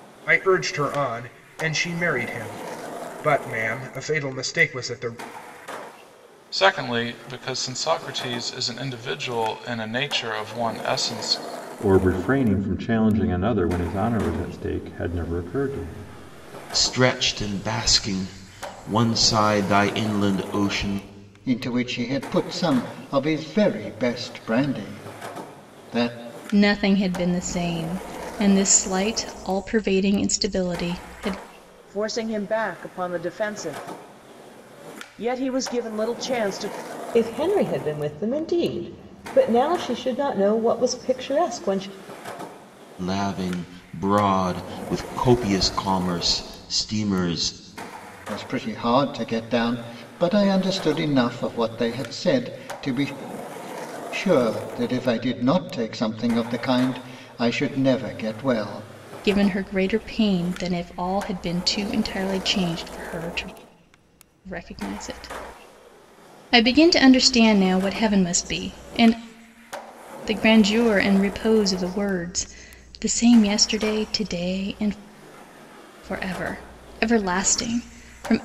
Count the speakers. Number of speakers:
8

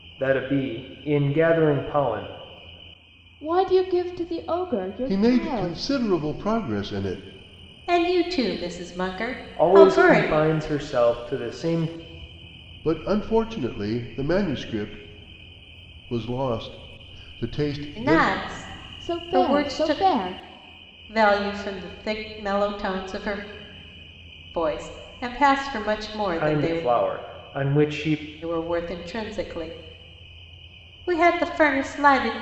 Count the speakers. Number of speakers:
4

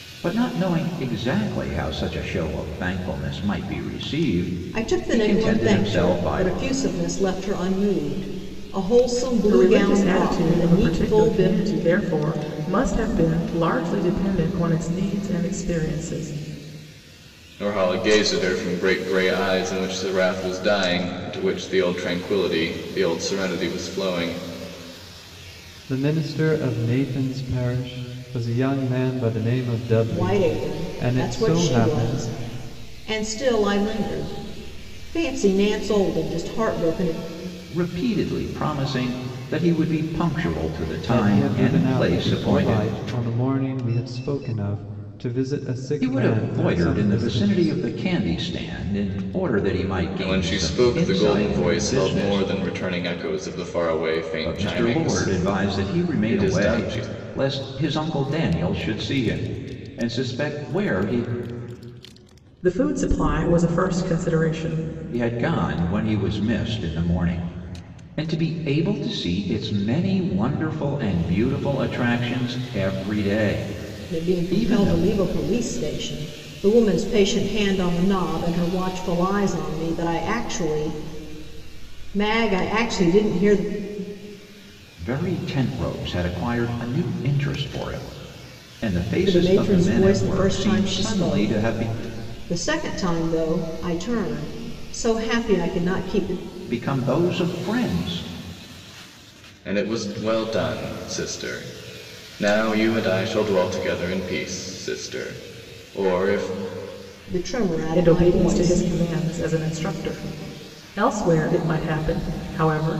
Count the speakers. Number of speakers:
5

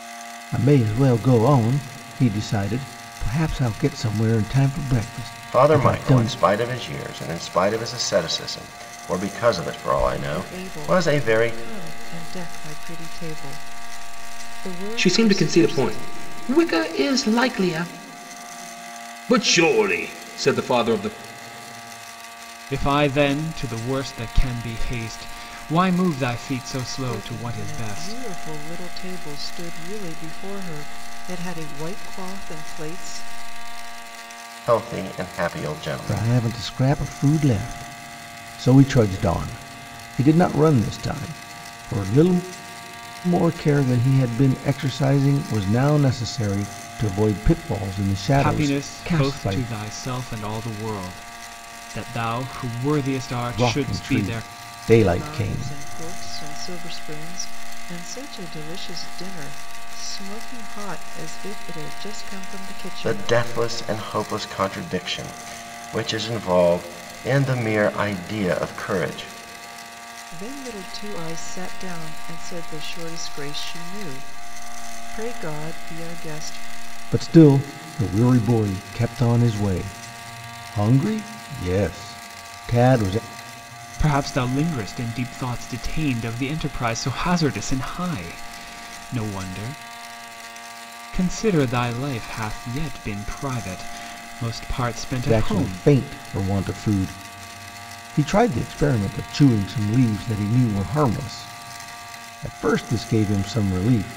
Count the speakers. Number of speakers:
5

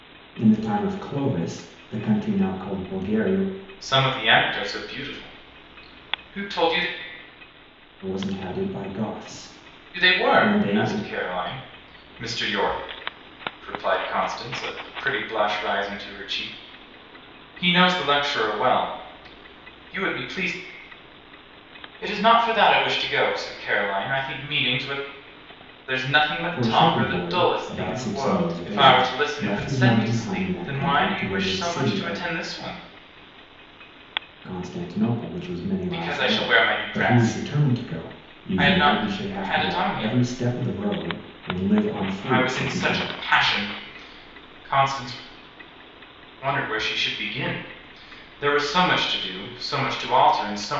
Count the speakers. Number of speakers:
2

